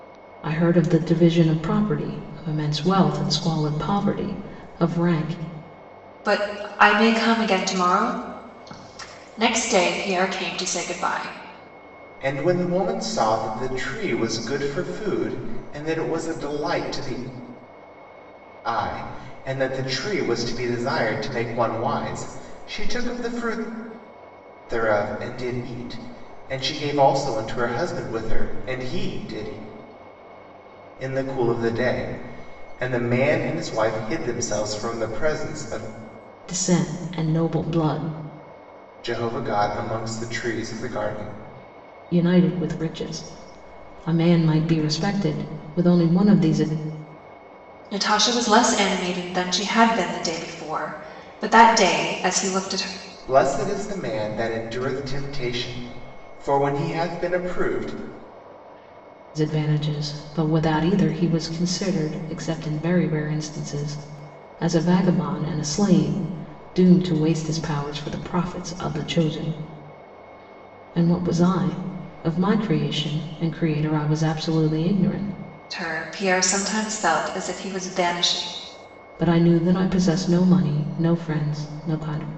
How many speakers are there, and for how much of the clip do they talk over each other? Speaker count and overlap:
3, no overlap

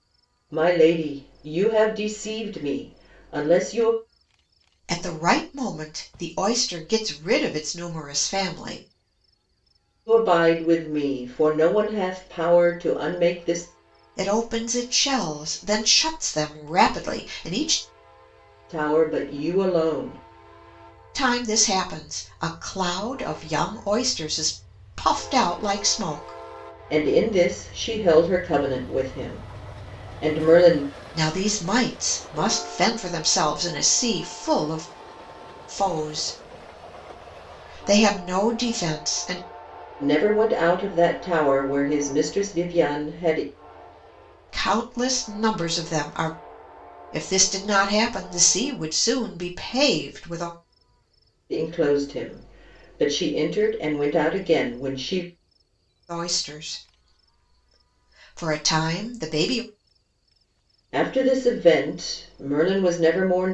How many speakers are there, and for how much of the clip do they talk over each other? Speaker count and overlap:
2, no overlap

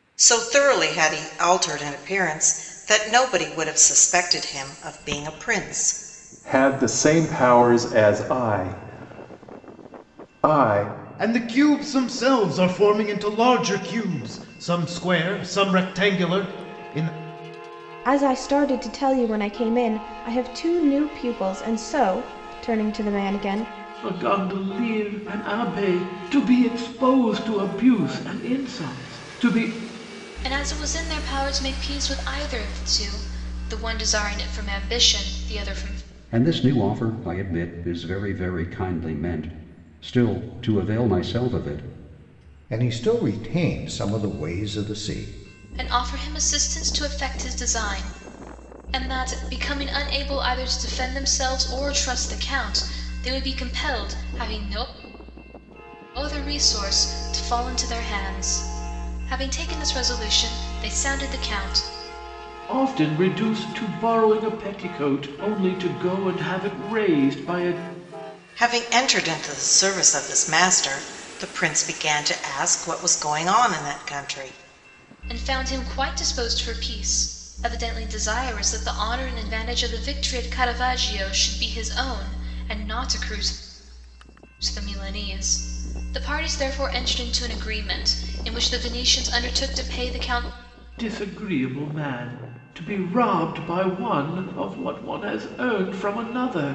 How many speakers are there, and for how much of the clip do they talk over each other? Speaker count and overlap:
8, no overlap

